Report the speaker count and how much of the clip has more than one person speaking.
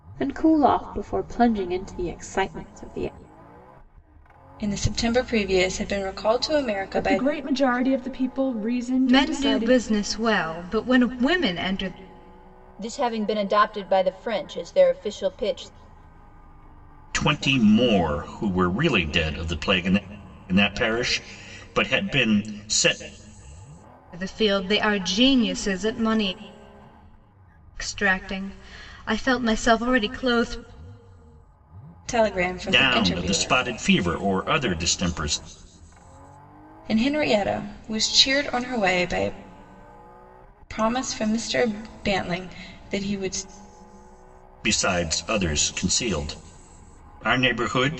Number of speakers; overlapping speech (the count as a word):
six, about 5%